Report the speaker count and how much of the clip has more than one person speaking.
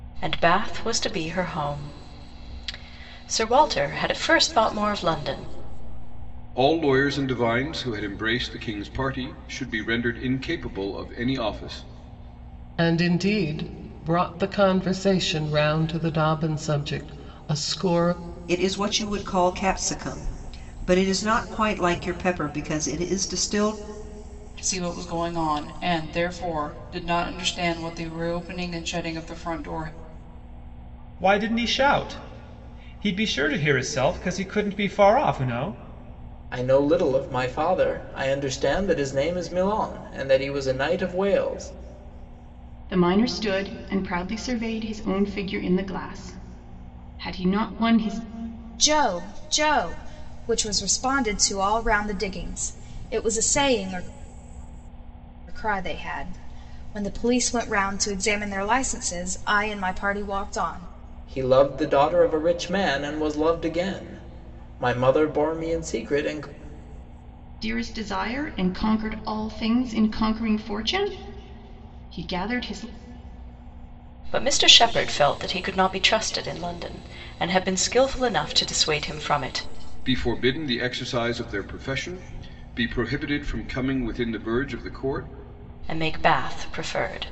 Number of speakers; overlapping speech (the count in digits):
9, no overlap